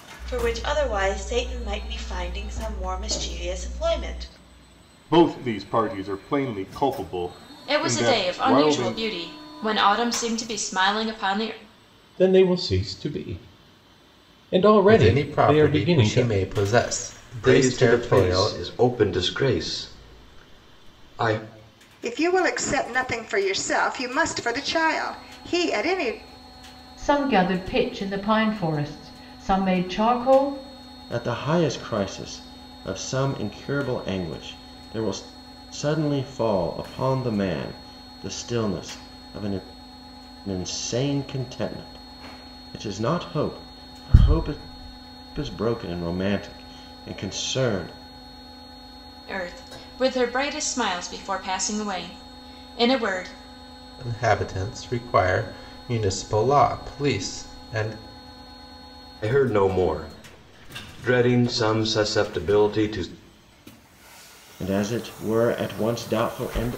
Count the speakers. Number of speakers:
9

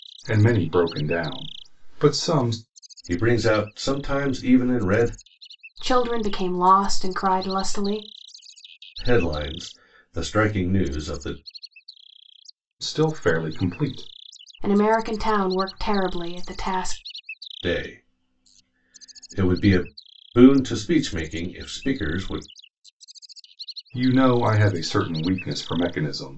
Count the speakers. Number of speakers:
3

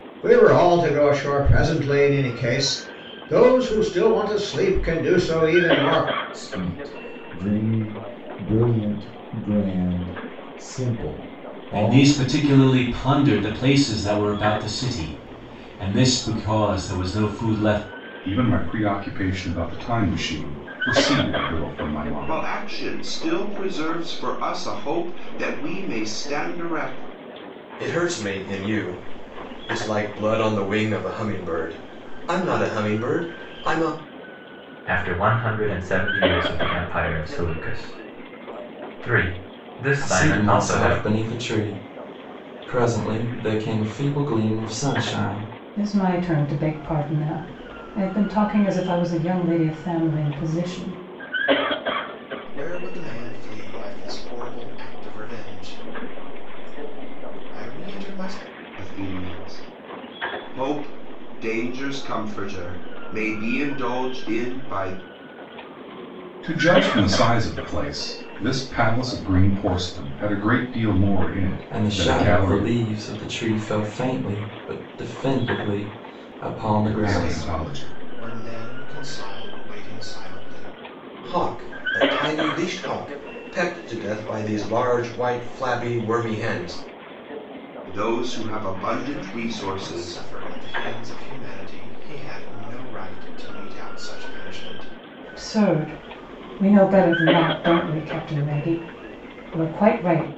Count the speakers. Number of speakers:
10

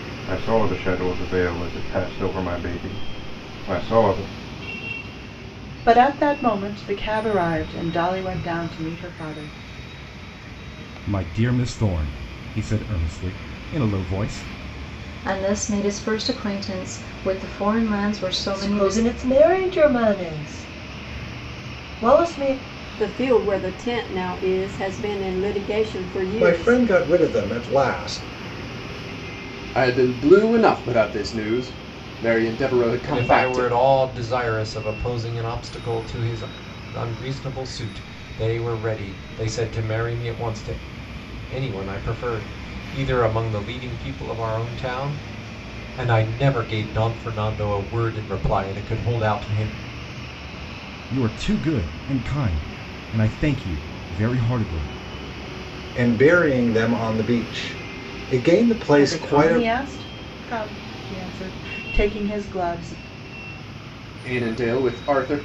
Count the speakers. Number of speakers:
9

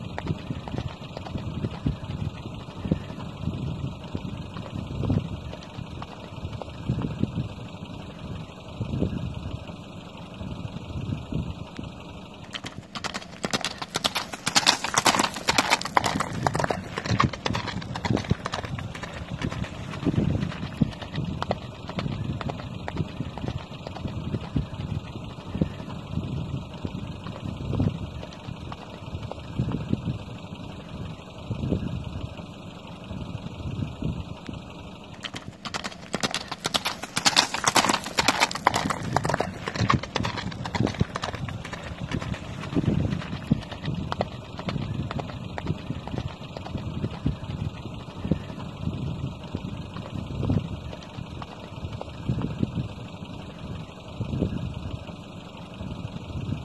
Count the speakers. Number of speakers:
0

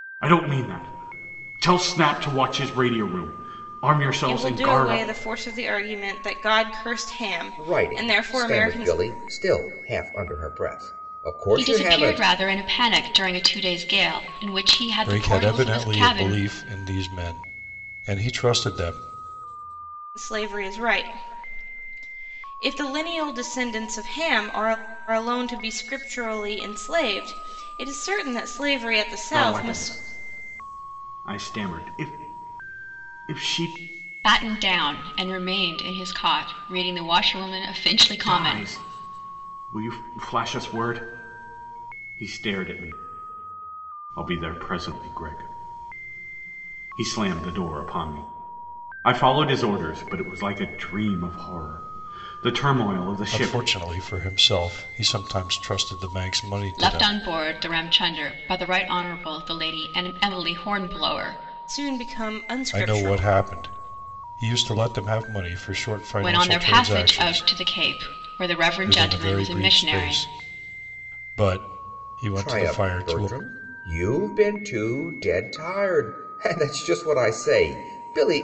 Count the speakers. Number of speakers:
5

